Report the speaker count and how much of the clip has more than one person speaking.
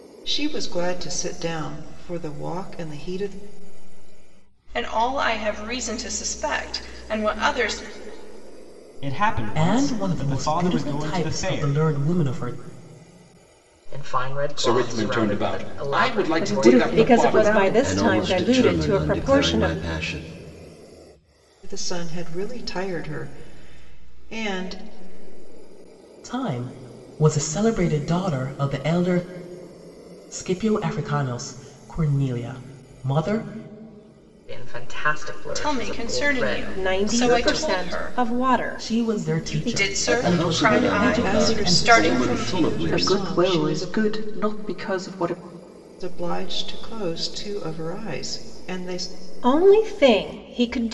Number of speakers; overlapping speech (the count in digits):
9, about 30%